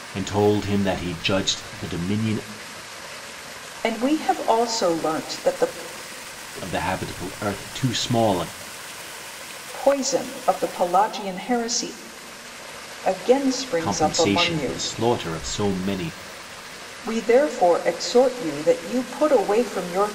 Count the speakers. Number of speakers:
2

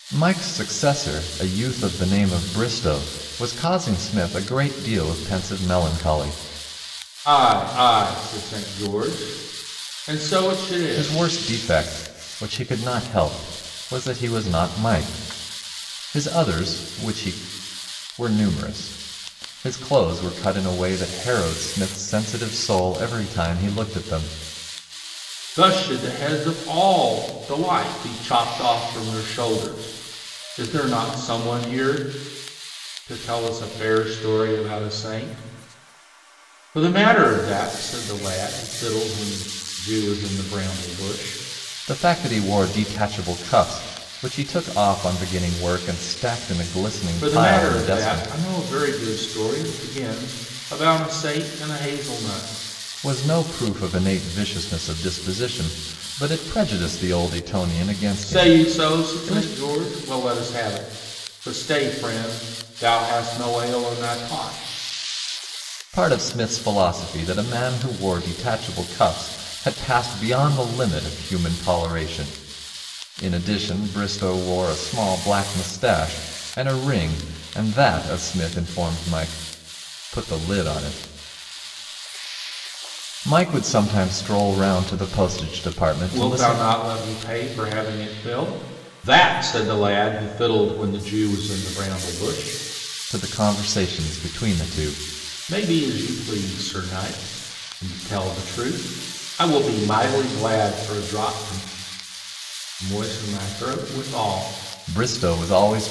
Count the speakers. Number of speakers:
2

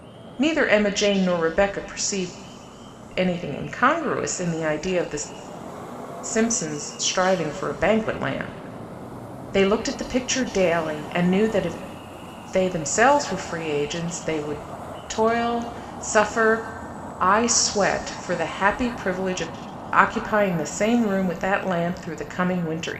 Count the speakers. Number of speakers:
1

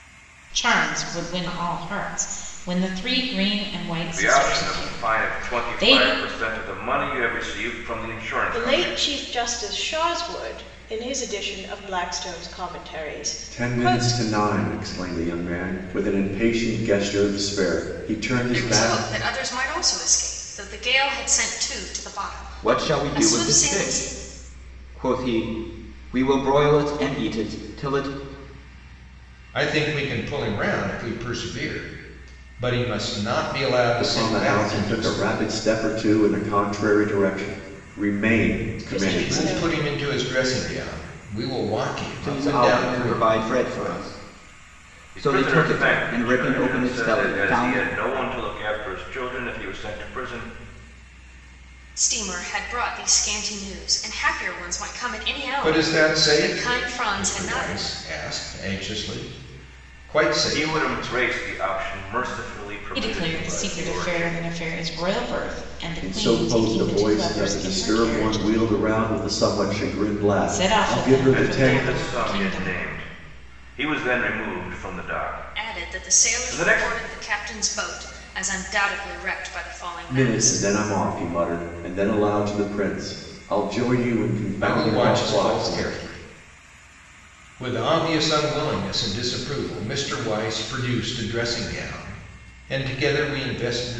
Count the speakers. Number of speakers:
7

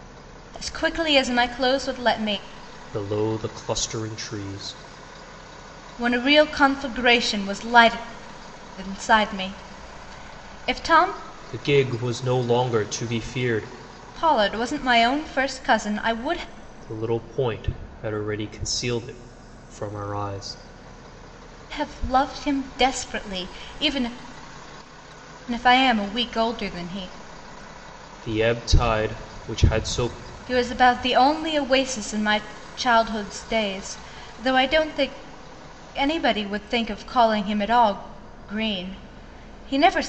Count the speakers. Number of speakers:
2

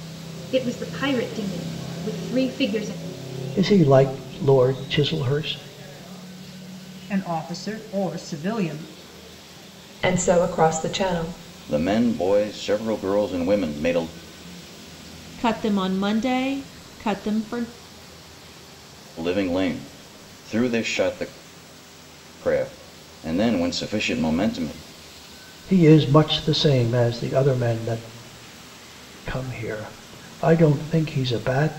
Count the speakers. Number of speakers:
6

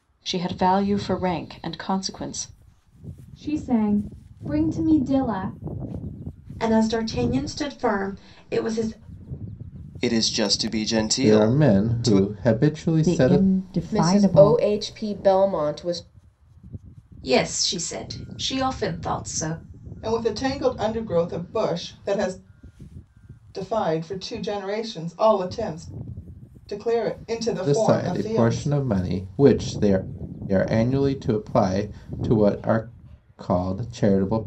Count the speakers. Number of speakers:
9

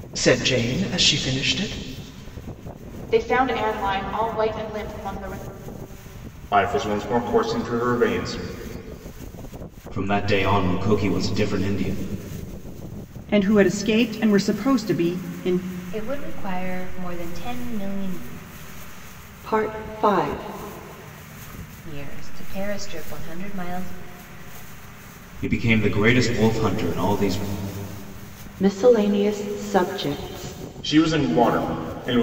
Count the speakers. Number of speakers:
7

